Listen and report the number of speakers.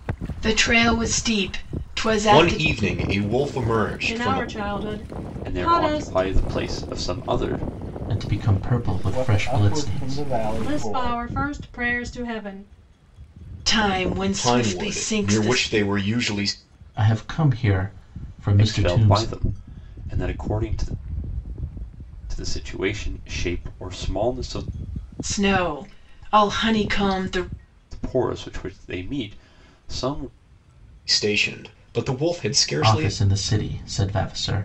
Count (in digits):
6